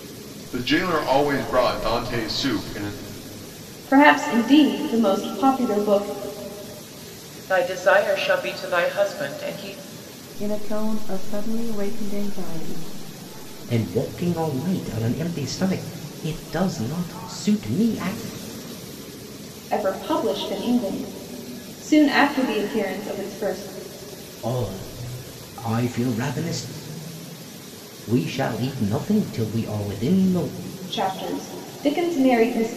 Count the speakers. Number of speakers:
5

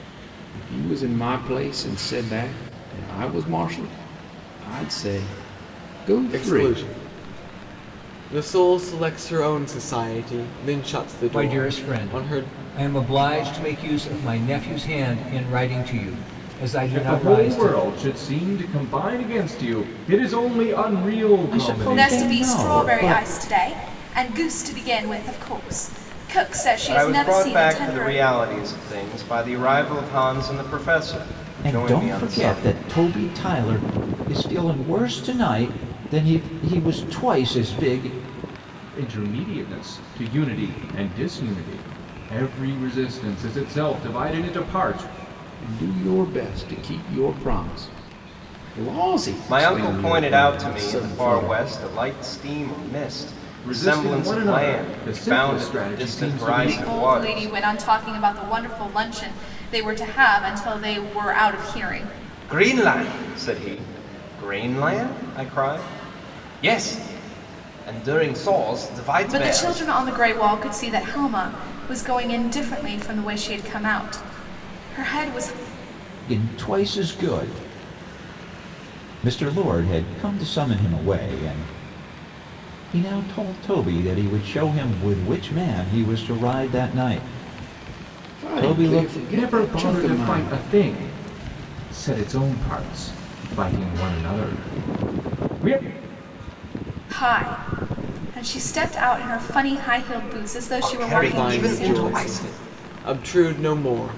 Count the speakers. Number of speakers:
7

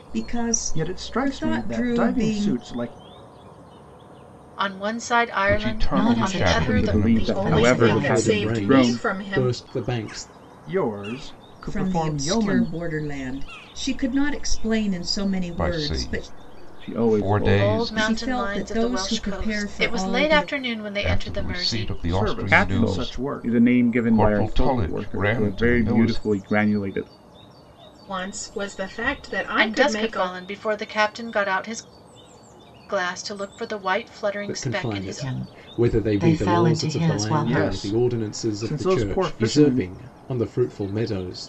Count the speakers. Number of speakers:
8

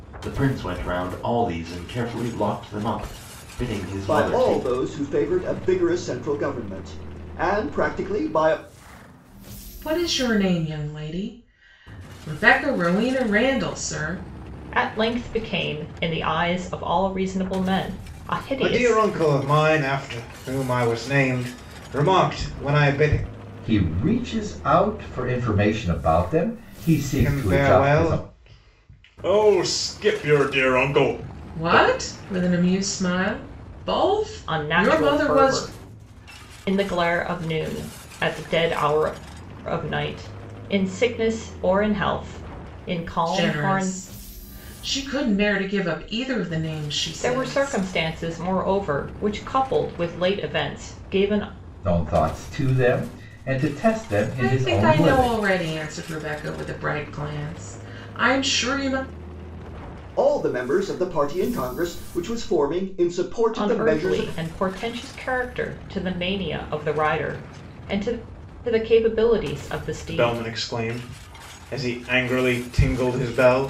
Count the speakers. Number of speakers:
6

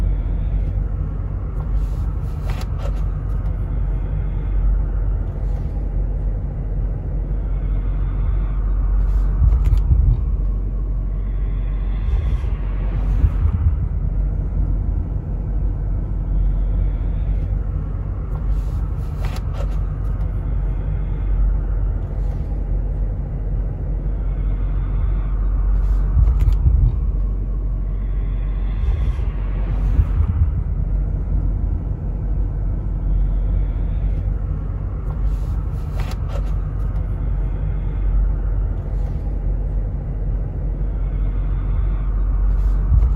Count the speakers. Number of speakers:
0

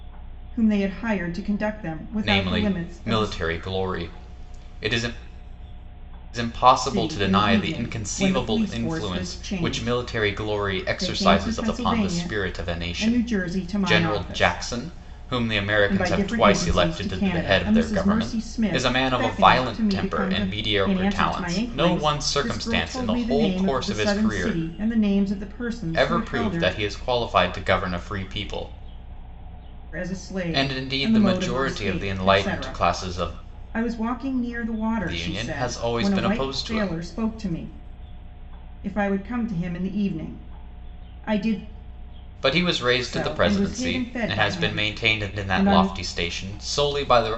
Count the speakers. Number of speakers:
2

